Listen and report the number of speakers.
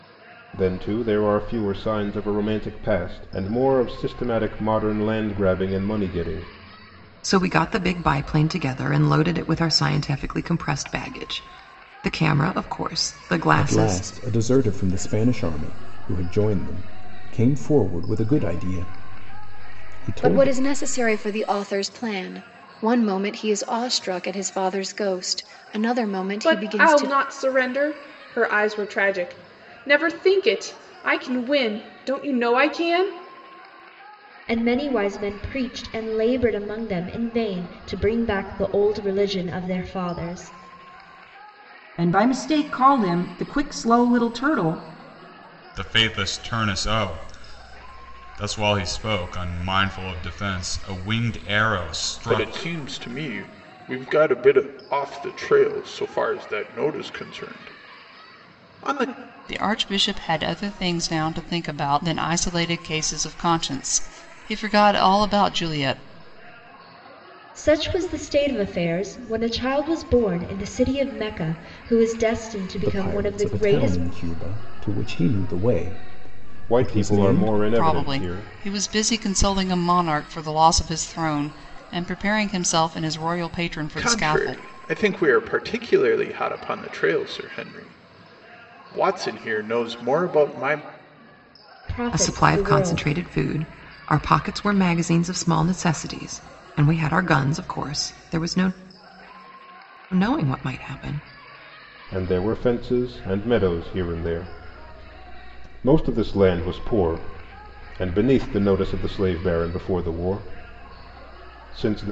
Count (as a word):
ten